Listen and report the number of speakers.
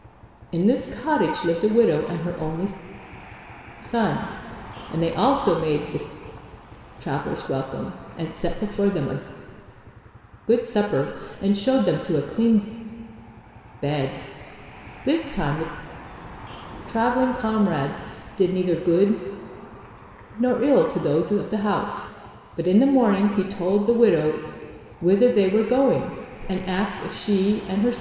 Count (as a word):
one